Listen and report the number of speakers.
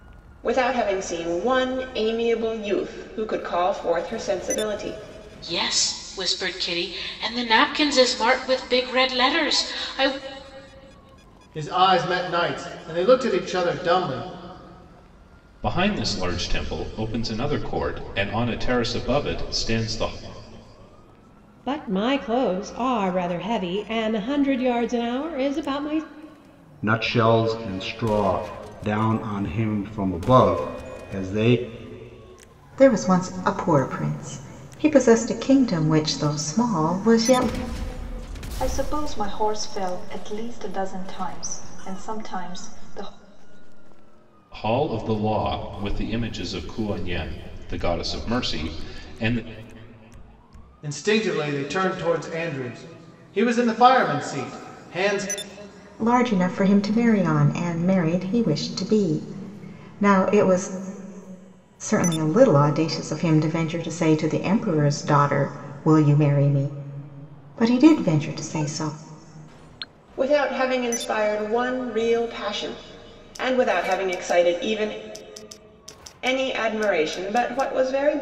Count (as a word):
eight